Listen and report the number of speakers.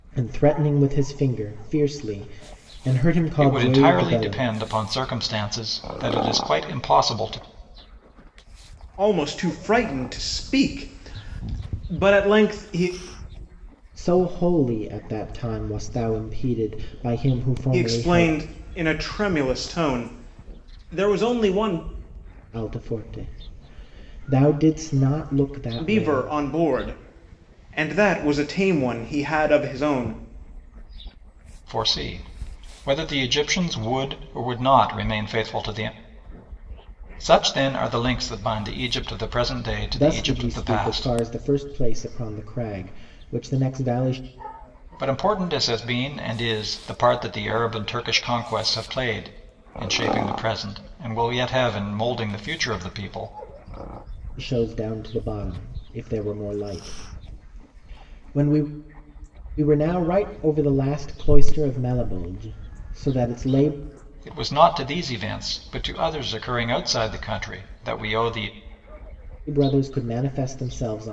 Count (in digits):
3